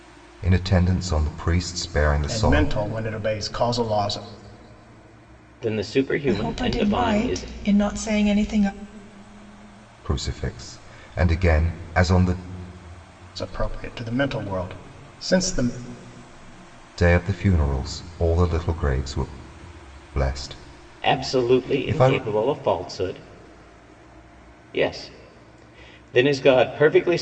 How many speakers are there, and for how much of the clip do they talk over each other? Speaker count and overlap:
four, about 11%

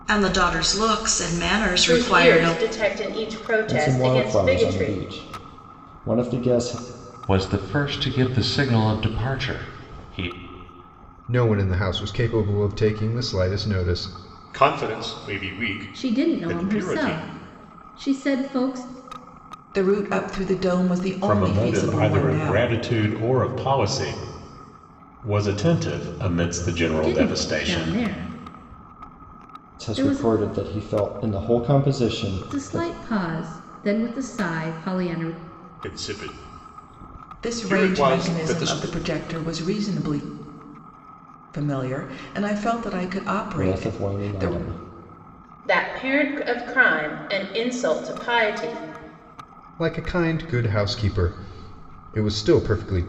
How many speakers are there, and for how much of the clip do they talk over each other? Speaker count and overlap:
nine, about 18%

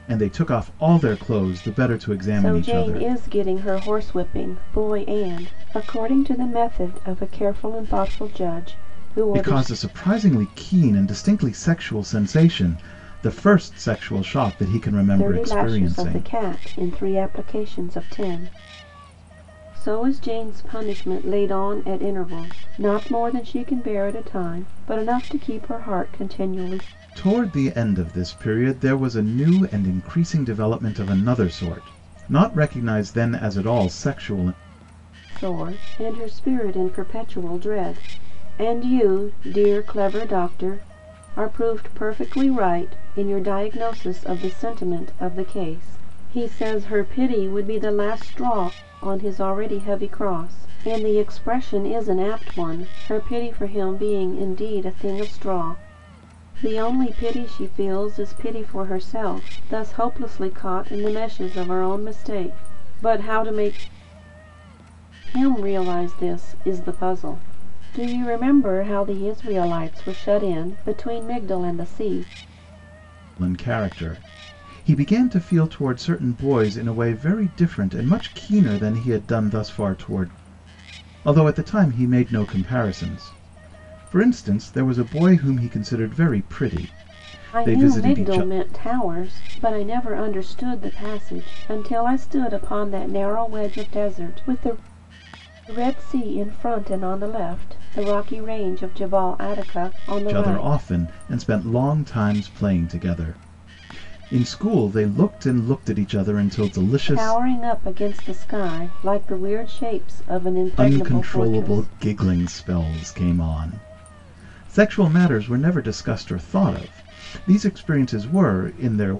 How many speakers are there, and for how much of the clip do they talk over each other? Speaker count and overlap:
two, about 4%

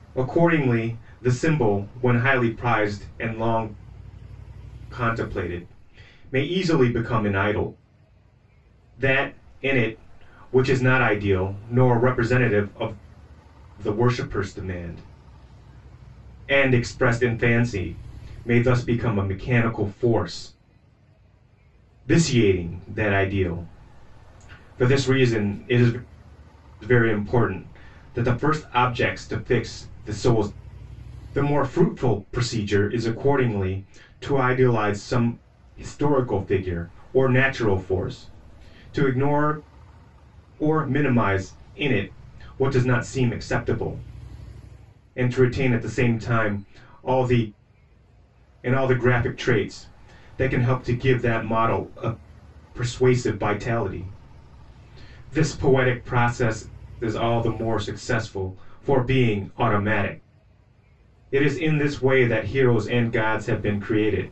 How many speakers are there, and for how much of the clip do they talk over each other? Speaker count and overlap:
one, no overlap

